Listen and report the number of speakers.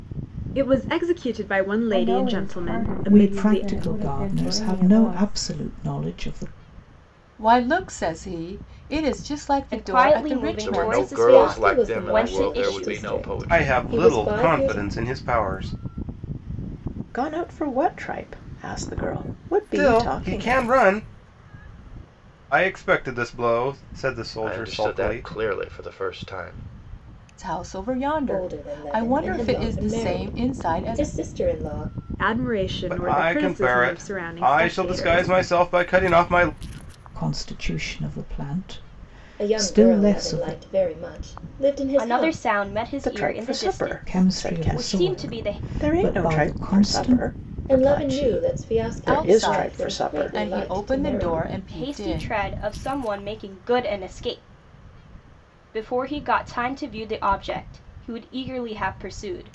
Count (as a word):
nine